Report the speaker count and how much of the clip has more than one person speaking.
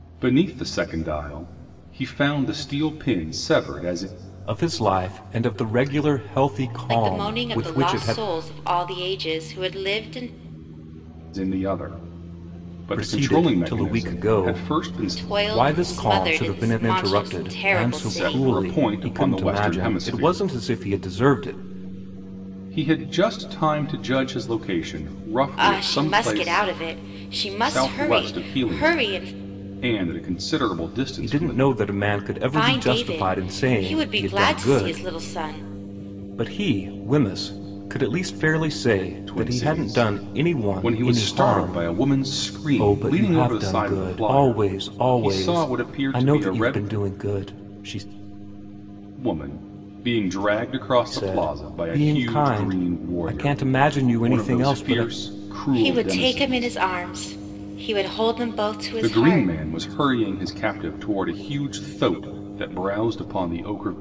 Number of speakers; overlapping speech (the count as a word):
three, about 44%